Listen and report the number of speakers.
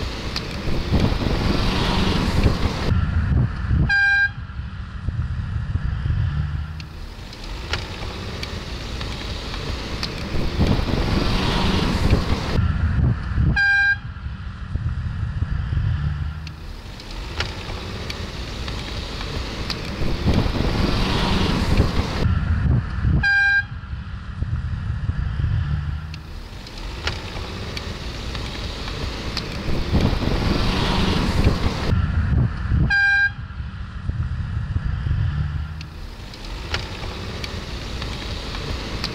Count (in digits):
0